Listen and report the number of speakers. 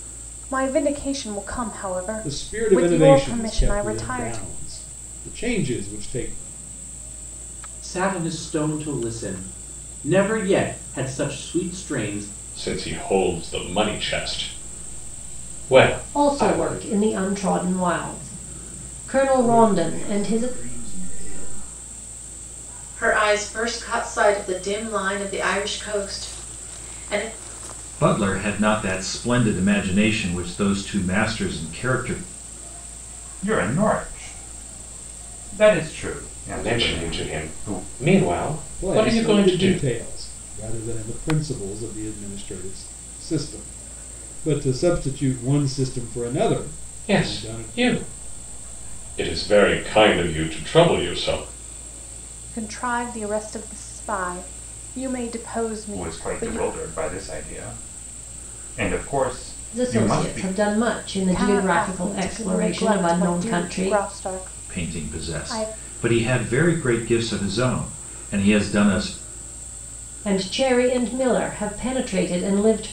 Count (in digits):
9